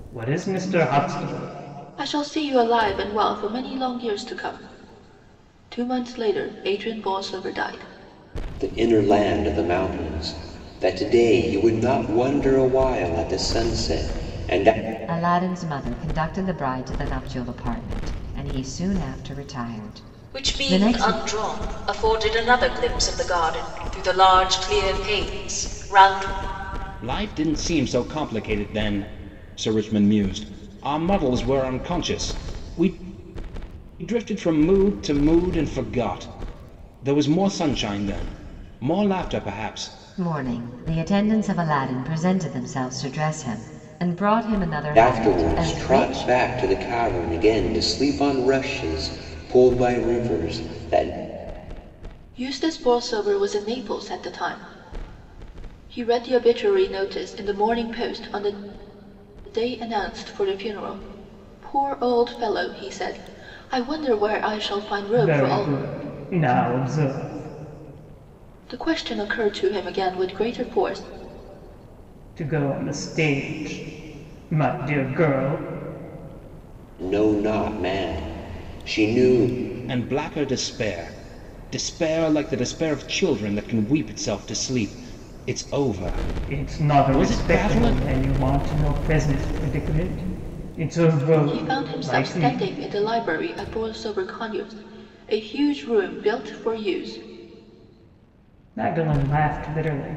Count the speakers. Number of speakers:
six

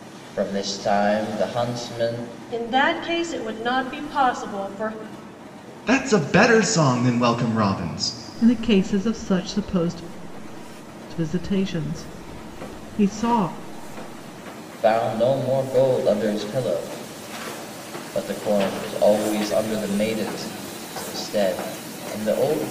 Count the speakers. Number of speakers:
four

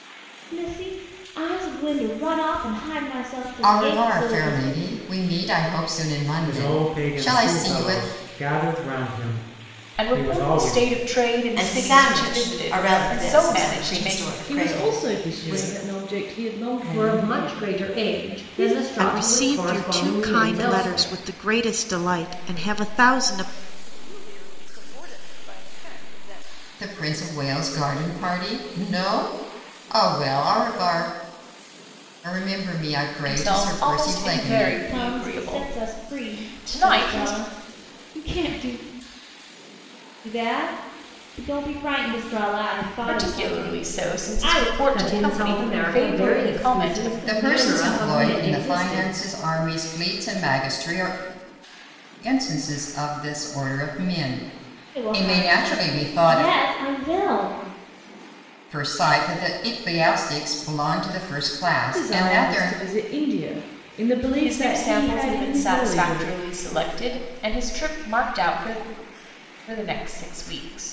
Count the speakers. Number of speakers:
nine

